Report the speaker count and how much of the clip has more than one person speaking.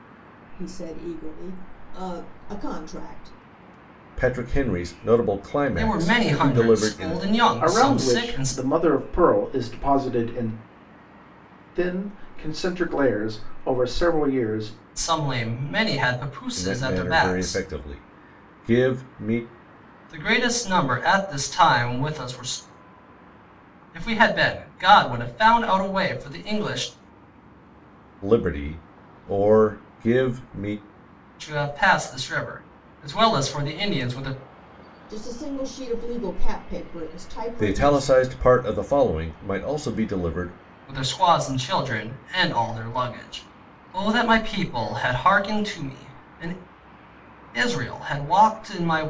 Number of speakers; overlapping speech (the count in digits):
4, about 8%